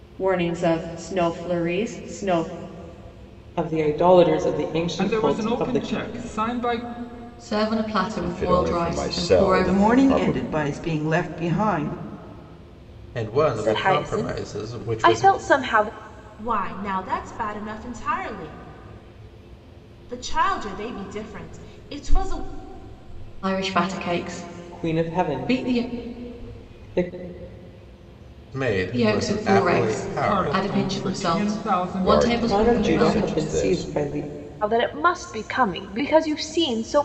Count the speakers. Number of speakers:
9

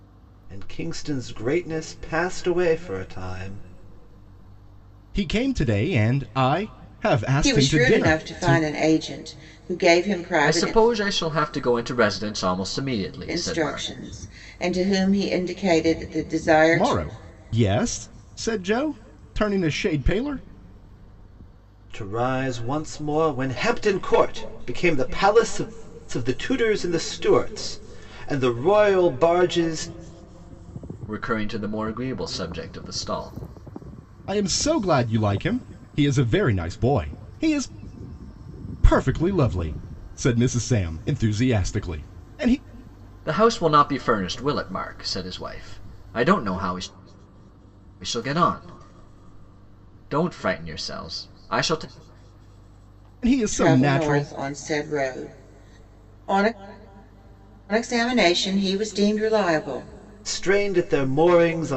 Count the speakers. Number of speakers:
4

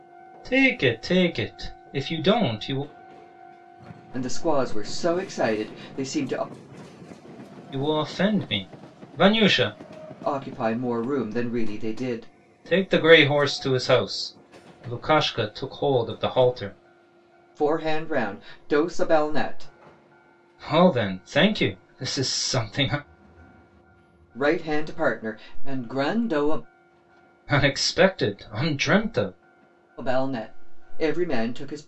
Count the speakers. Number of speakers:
2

